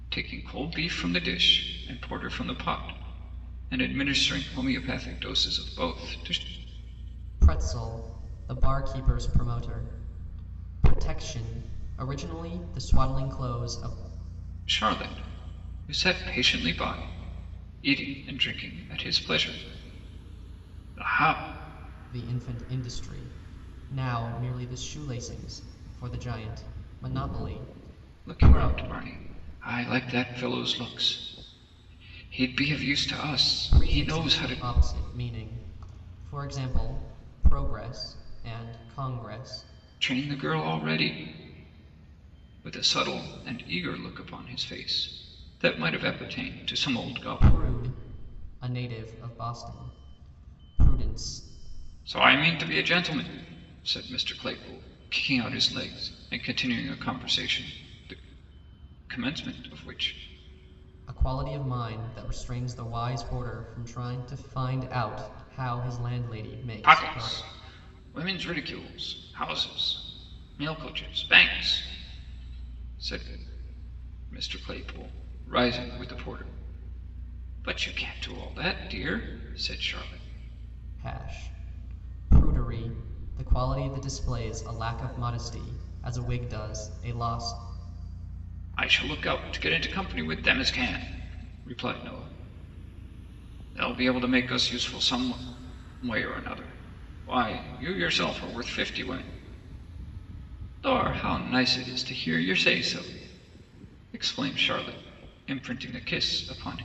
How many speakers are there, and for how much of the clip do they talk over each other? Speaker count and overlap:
2, about 2%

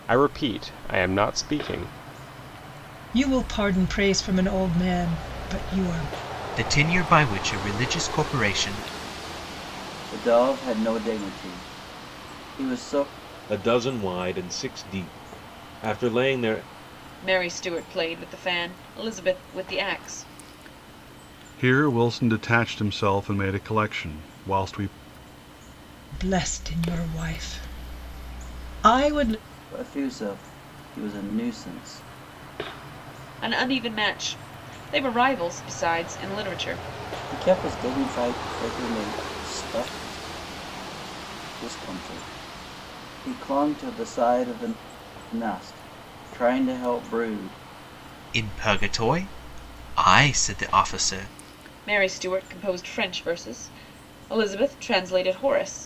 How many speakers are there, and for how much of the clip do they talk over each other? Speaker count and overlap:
7, no overlap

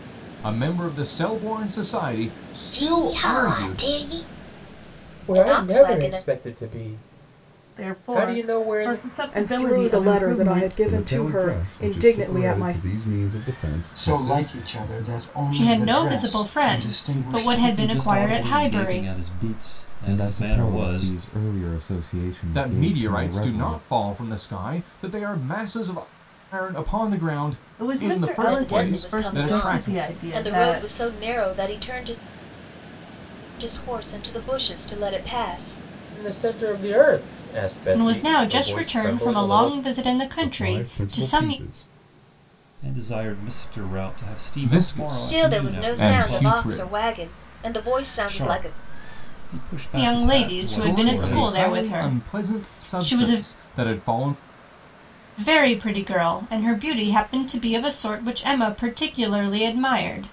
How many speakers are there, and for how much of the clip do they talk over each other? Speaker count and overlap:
10, about 44%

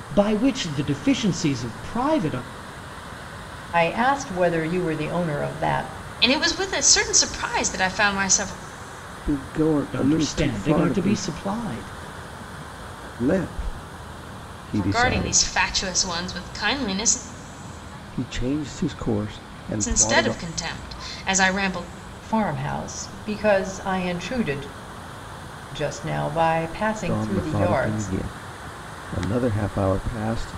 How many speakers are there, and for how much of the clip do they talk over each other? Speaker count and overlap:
4, about 12%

